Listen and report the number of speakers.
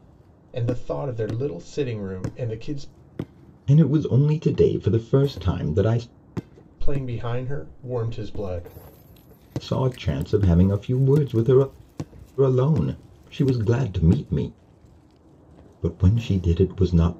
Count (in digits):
2